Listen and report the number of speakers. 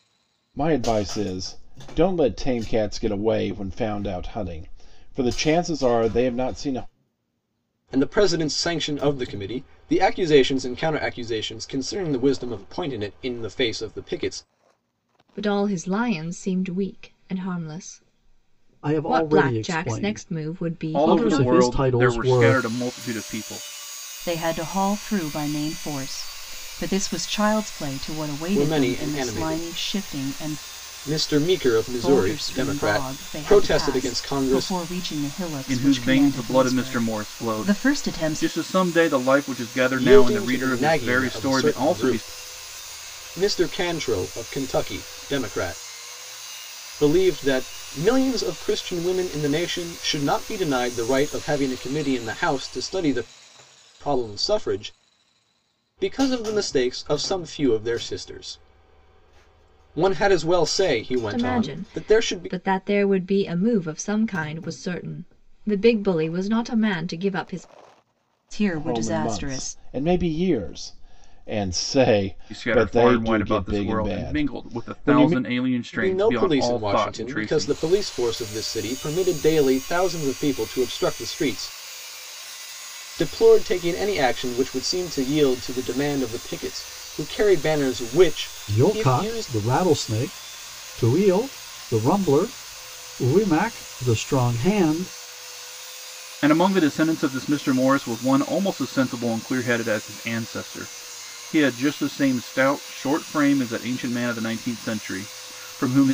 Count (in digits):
6